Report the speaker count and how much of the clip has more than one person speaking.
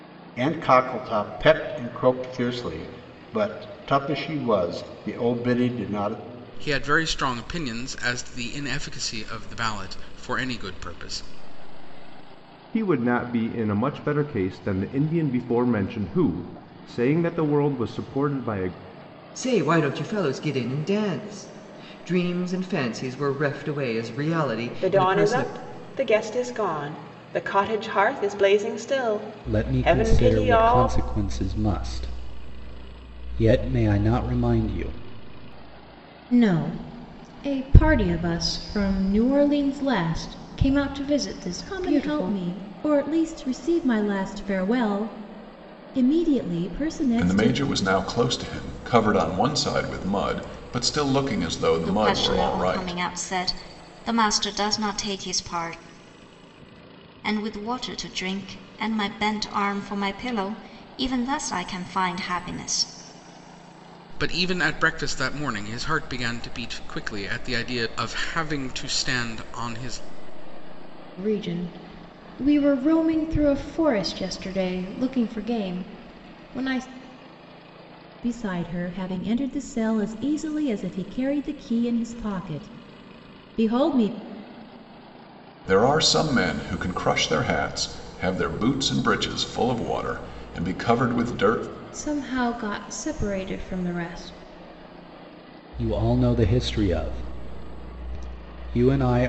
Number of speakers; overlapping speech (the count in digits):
10, about 5%